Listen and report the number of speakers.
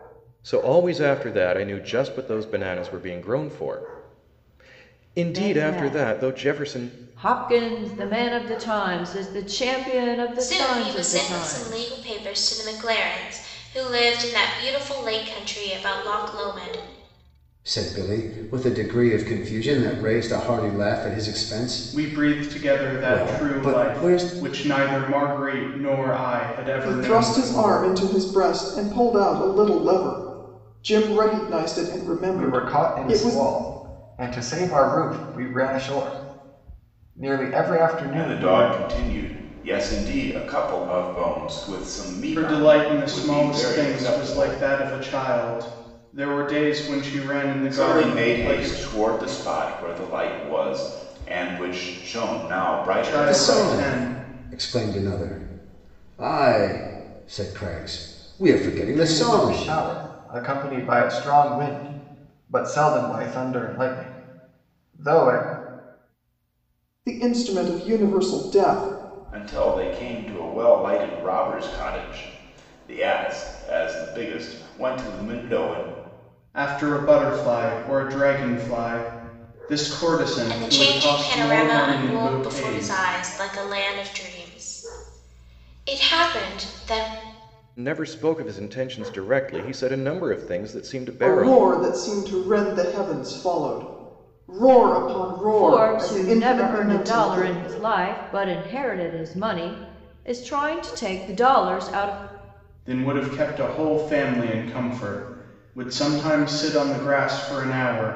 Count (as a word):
eight